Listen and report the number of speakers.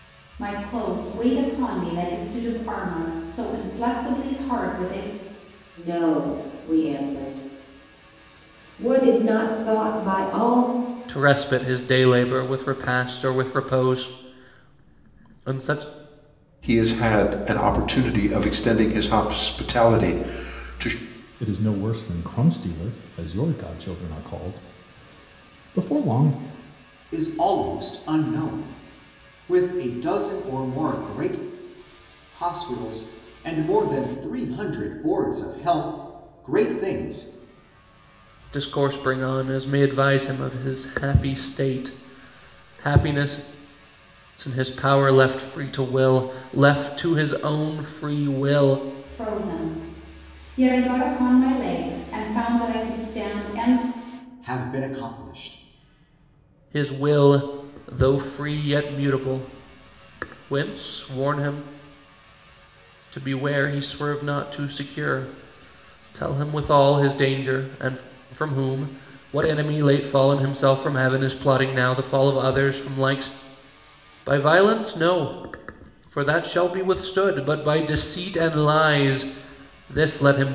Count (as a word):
six